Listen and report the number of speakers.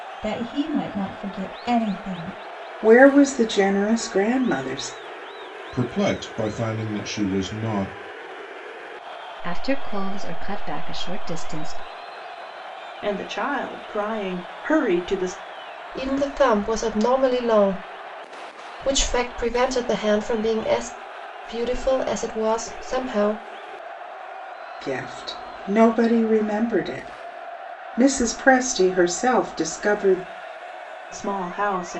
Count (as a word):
six